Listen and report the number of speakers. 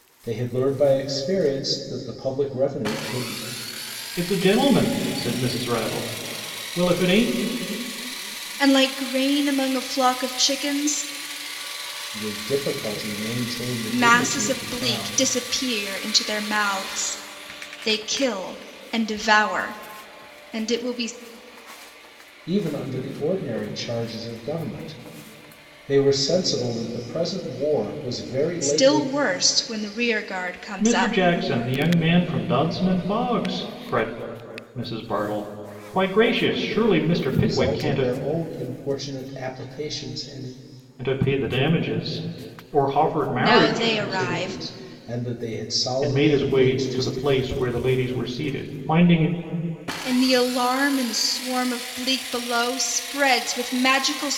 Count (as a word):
three